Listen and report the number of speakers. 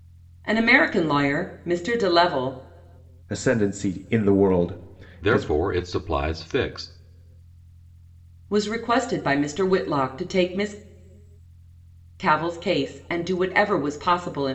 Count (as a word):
three